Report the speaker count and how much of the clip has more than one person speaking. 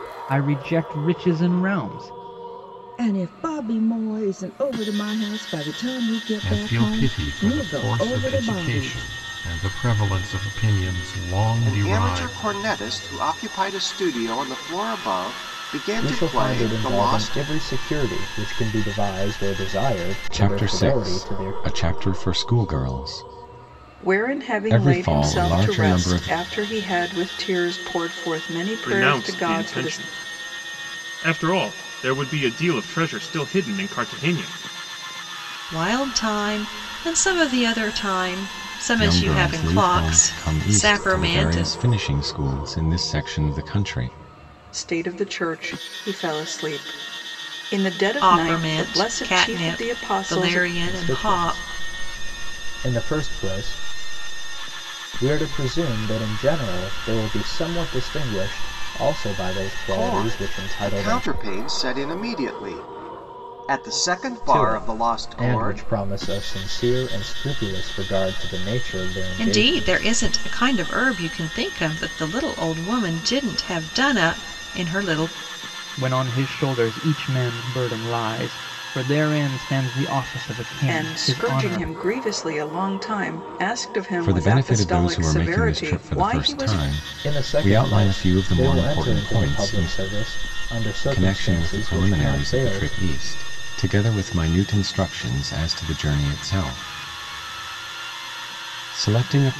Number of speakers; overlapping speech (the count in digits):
9, about 28%